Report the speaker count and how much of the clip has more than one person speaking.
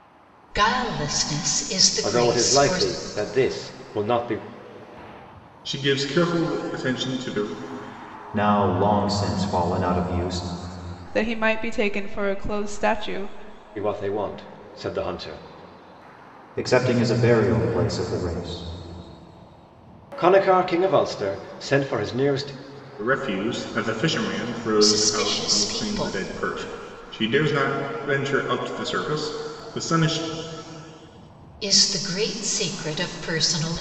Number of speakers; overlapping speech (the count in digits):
5, about 7%